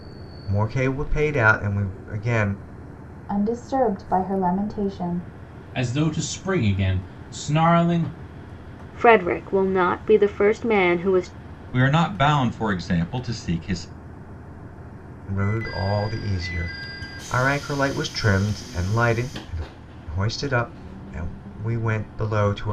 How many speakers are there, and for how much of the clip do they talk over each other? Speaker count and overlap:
5, no overlap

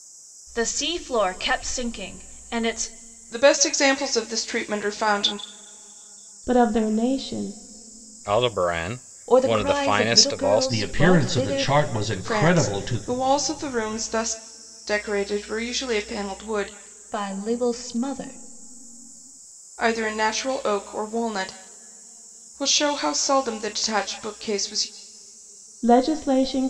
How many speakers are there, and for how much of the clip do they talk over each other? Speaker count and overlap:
6, about 12%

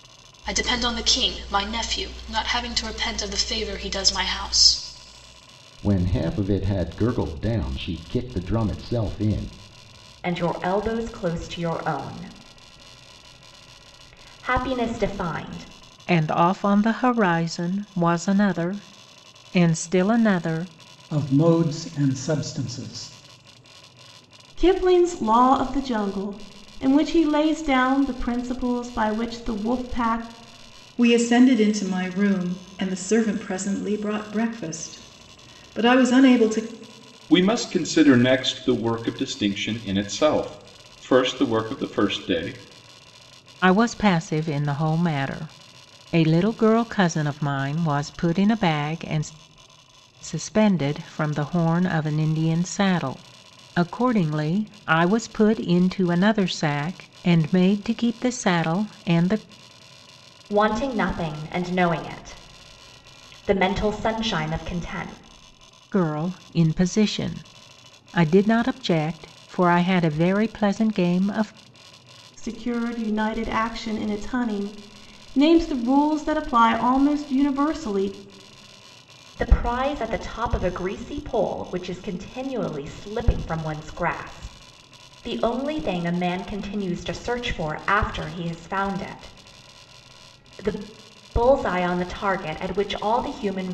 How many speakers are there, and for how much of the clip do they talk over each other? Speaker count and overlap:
8, no overlap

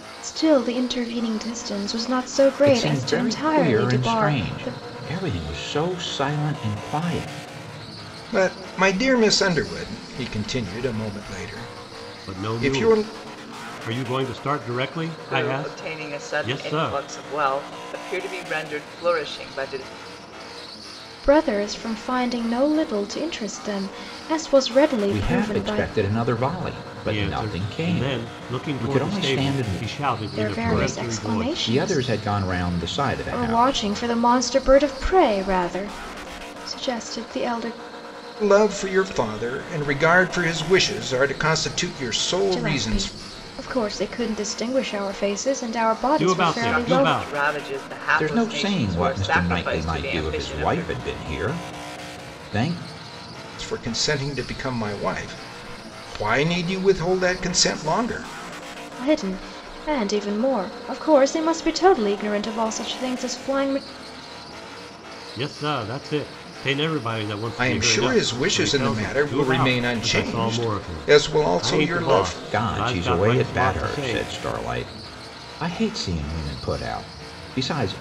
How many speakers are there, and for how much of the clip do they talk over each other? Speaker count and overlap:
5, about 29%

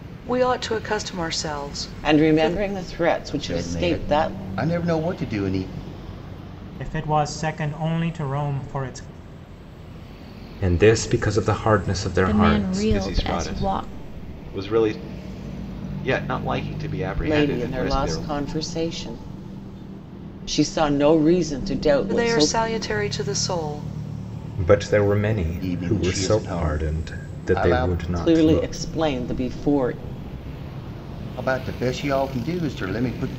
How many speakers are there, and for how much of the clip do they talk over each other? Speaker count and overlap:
7, about 24%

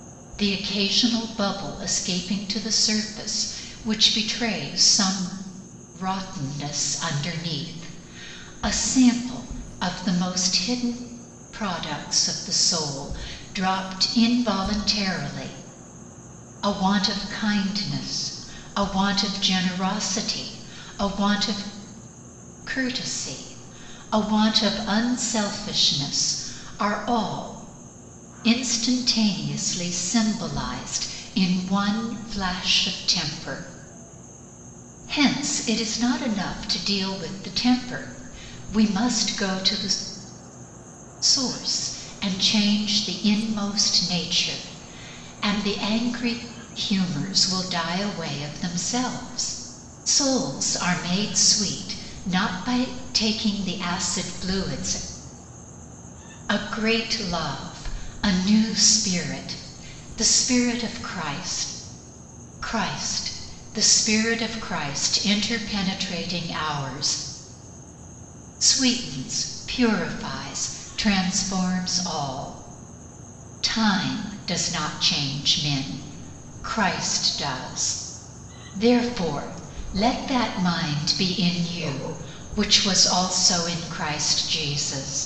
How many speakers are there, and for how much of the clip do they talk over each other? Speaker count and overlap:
1, no overlap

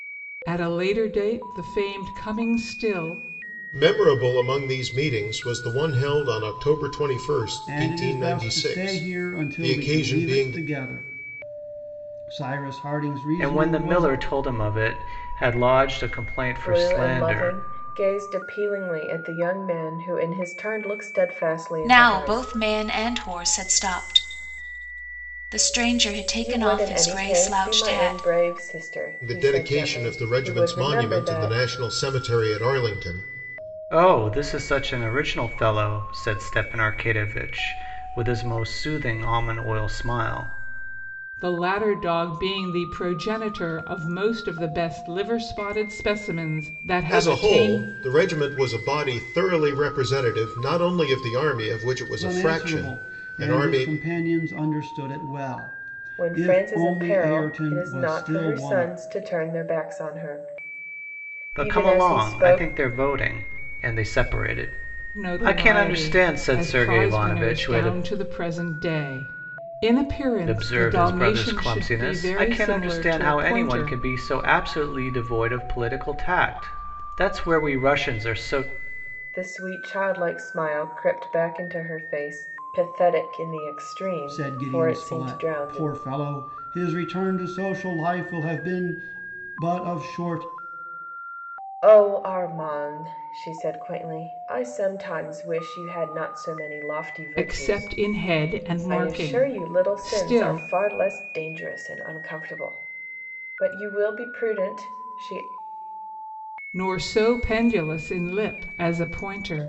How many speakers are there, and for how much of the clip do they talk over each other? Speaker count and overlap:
6, about 24%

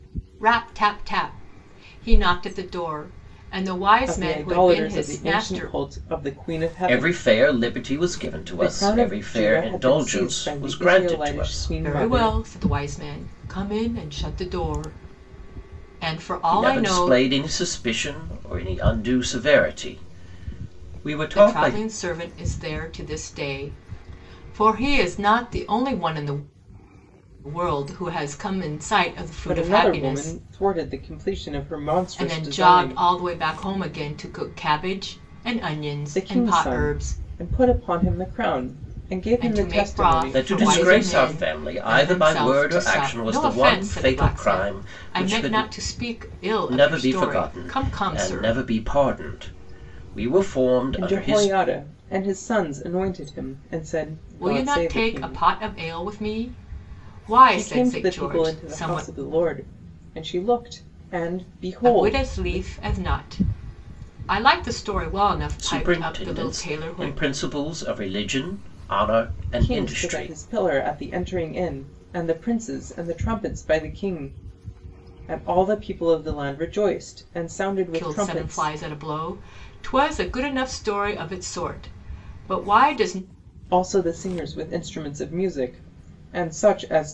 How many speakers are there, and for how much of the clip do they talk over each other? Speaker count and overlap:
3, about 31%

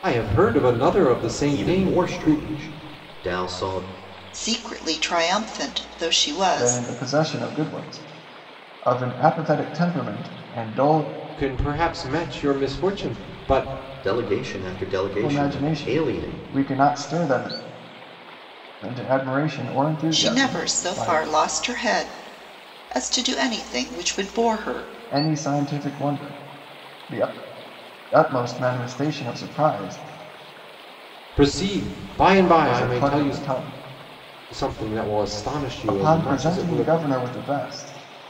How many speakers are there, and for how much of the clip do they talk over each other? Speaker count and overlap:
4, about 14%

